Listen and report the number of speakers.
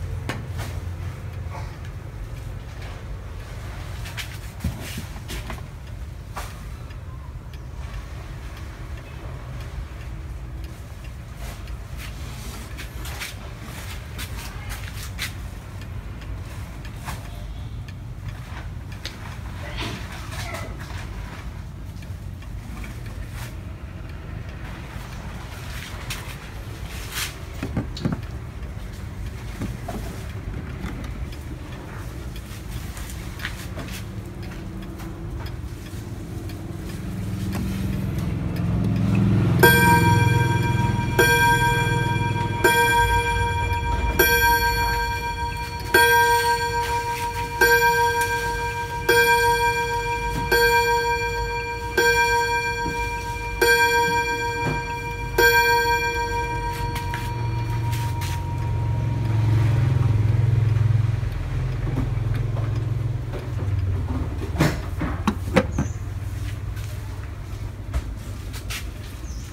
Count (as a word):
zero